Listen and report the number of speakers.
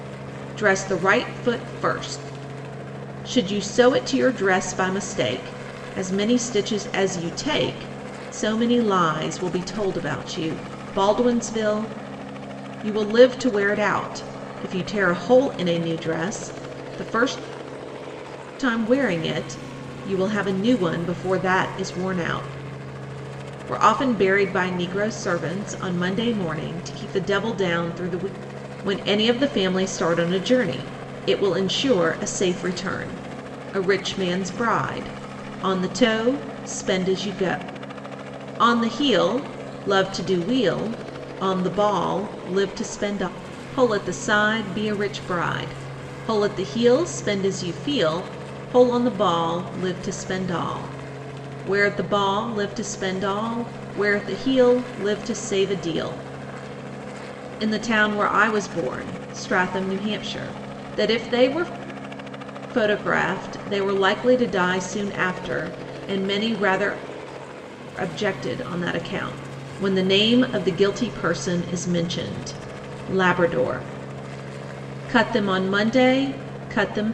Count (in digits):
1